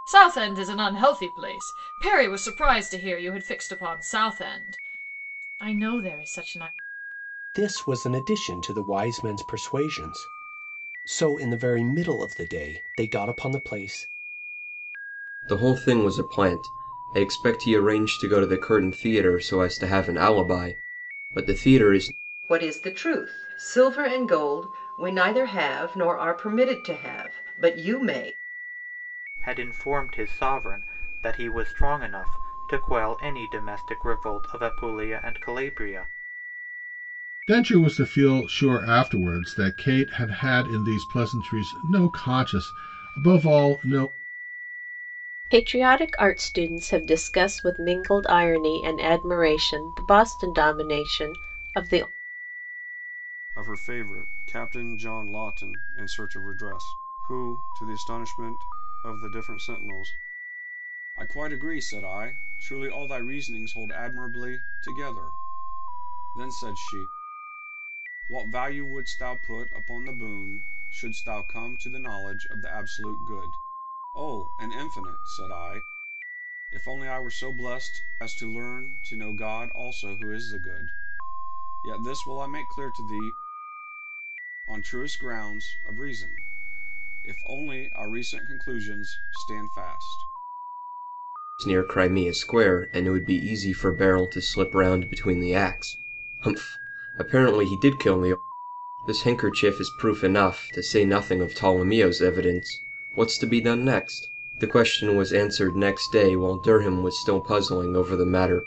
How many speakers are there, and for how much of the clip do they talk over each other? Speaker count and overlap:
8, no overlap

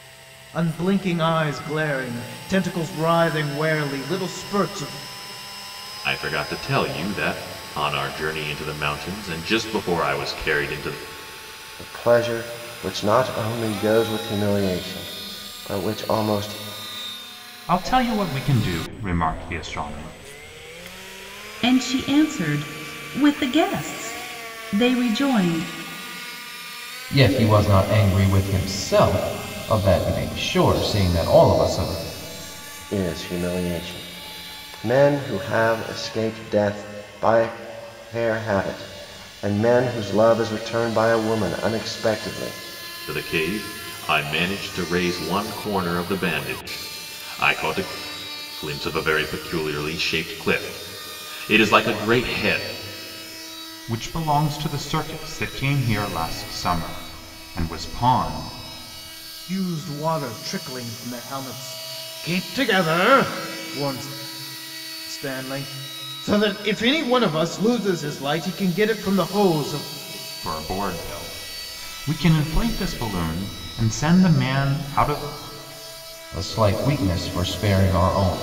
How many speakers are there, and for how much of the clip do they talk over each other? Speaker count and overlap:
6, no overlap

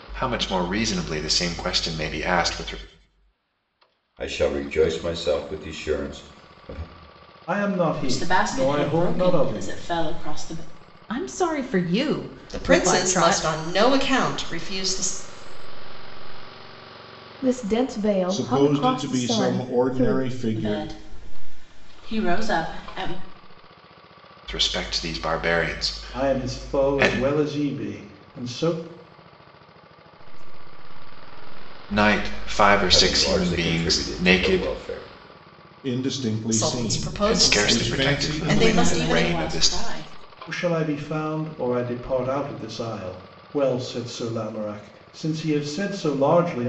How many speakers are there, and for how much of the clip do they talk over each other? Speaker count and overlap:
9, about 34%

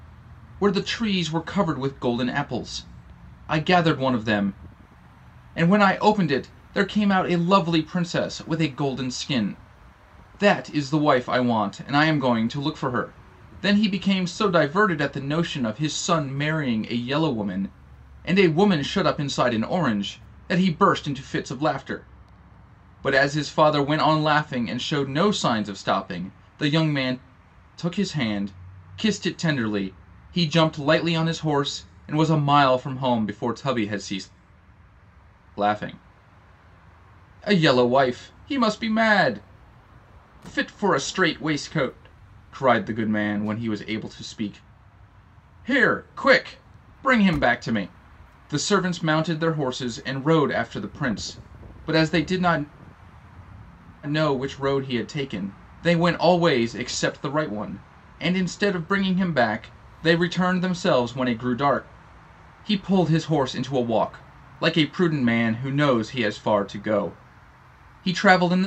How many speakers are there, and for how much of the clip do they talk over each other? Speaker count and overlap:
1, no overlap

